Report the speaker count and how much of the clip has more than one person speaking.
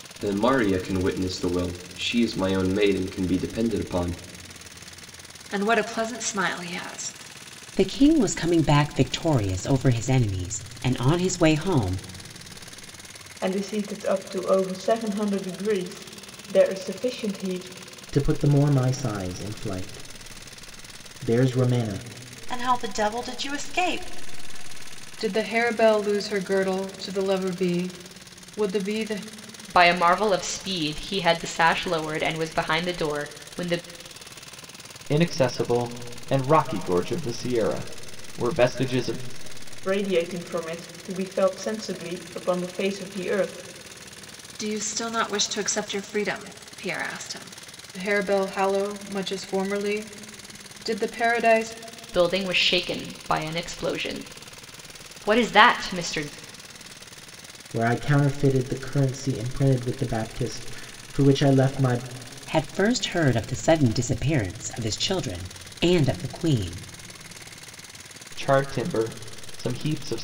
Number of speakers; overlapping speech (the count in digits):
9, no overlap